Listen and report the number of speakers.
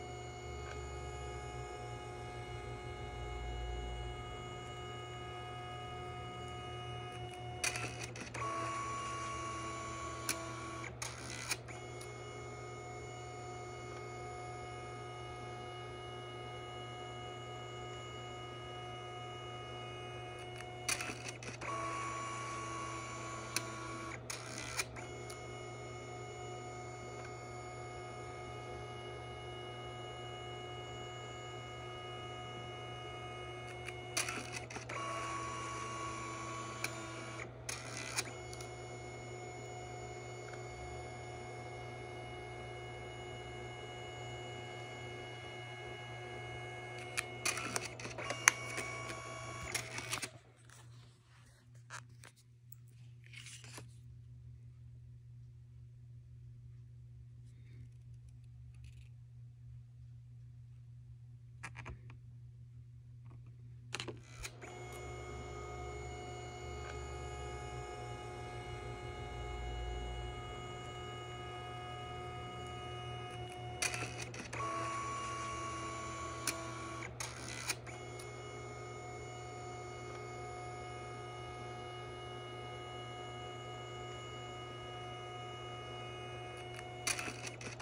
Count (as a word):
zero